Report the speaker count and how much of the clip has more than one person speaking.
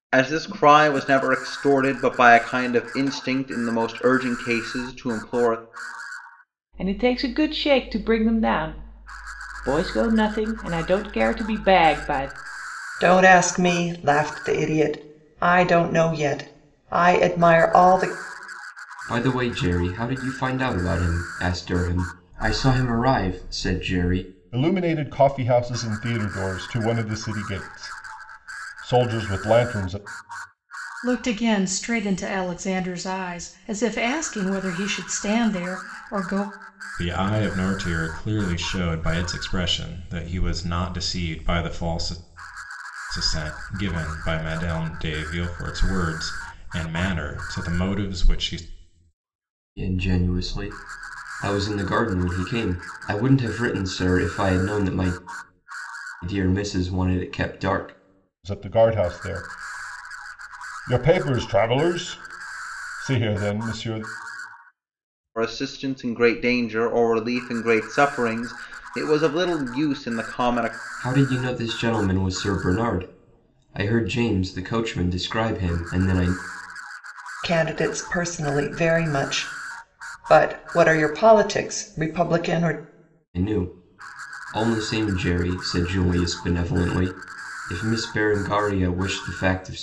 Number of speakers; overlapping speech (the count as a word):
seven, no overlap